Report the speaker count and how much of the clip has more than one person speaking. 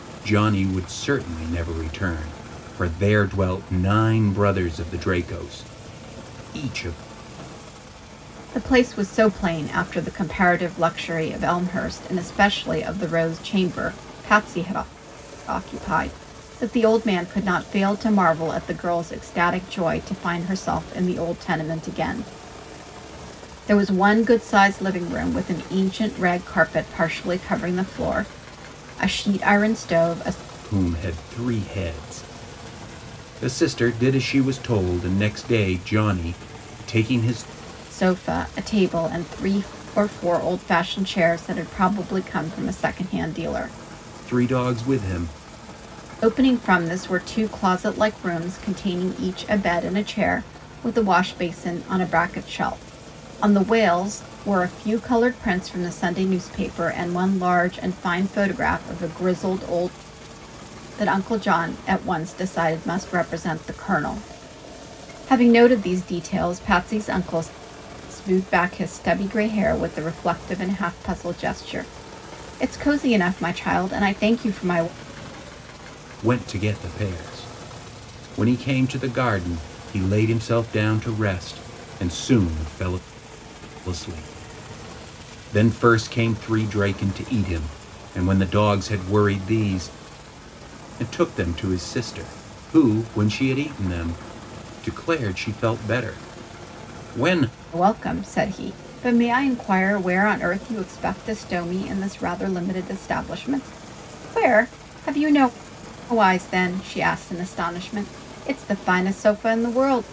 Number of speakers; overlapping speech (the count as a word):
two, no overlap